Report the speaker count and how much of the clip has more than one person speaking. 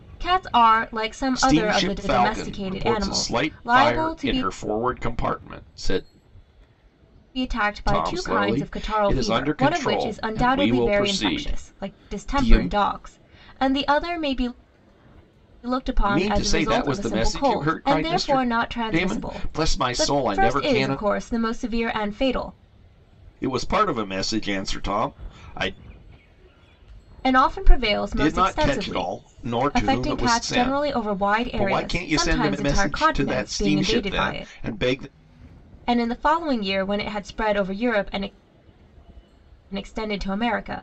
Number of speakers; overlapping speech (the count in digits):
2, about 45%